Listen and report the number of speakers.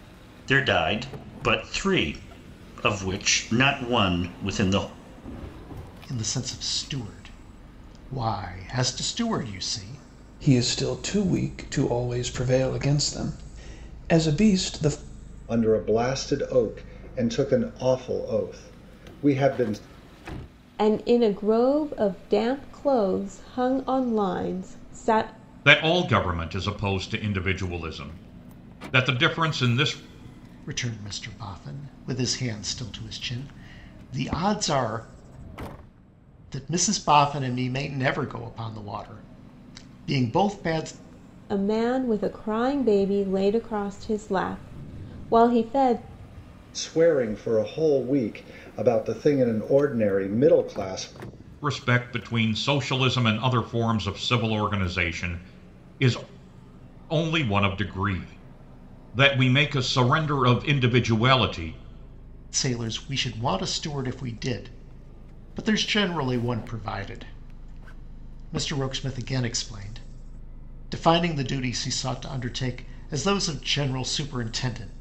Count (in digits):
6